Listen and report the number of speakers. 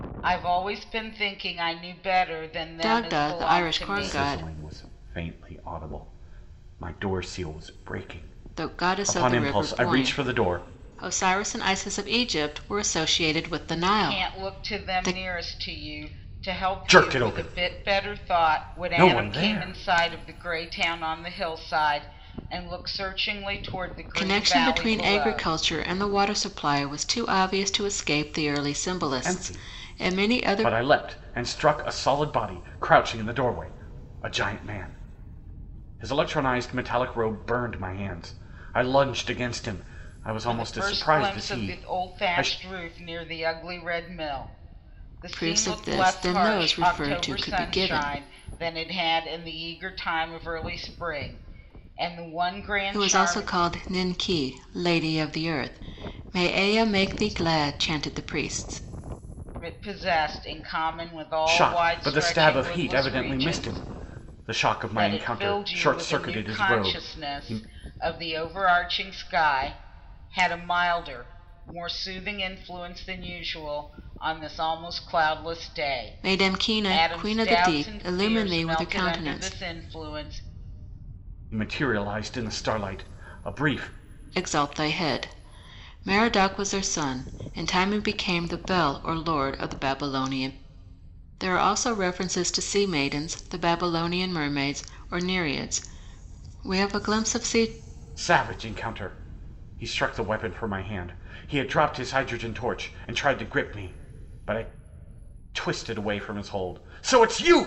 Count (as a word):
three